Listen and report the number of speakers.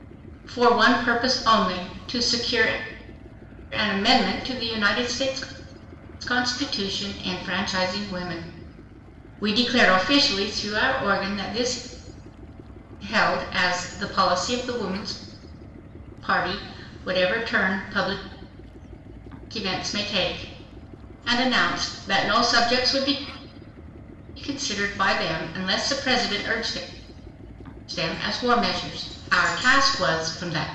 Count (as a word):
one